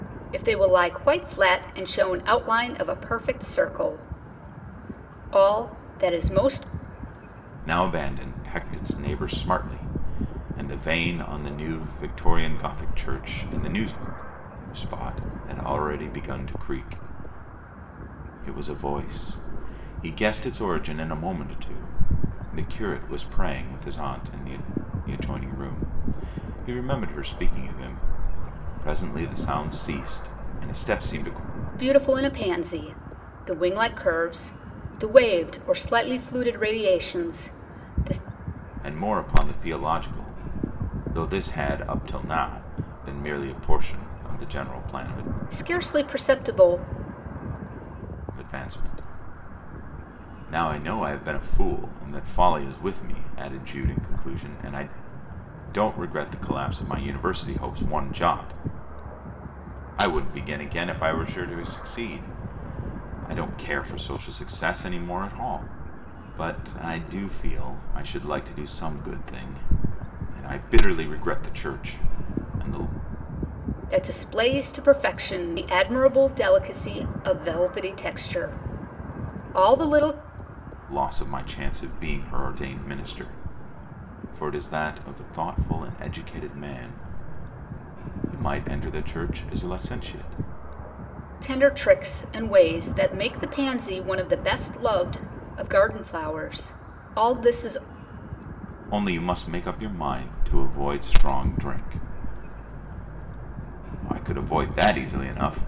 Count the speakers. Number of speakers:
2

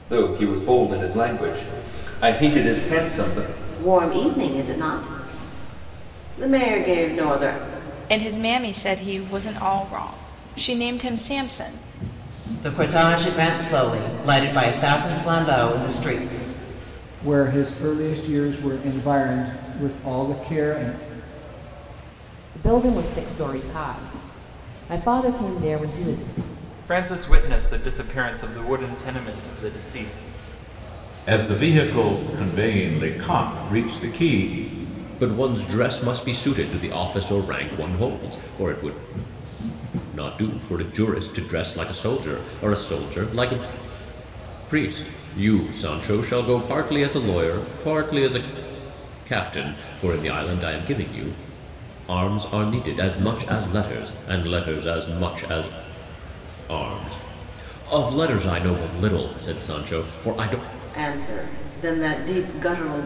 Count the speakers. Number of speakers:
9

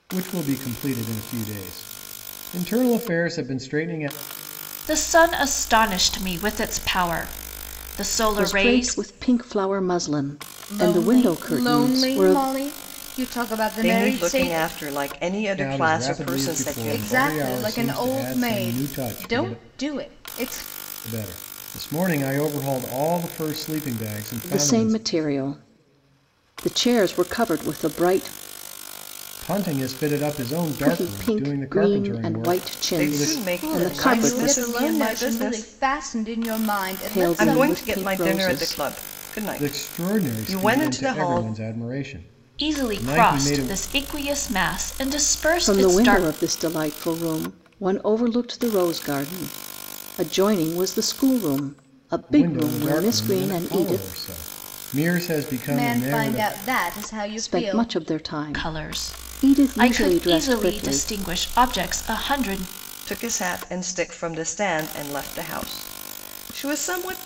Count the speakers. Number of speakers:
5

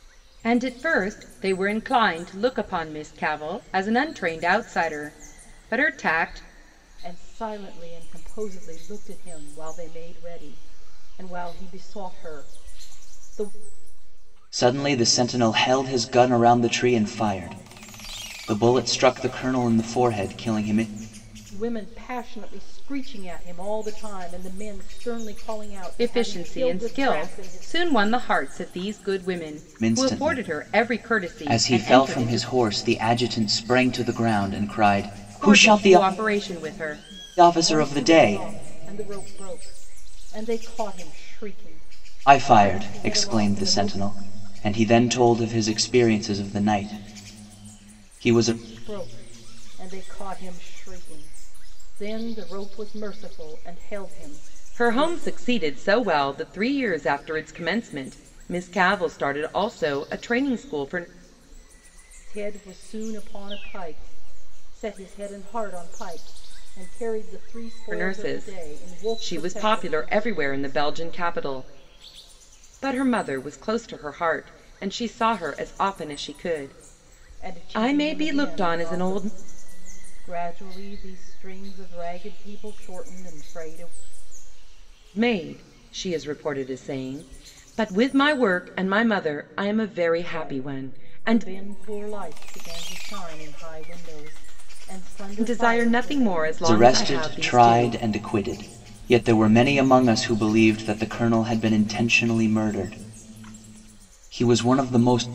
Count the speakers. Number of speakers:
3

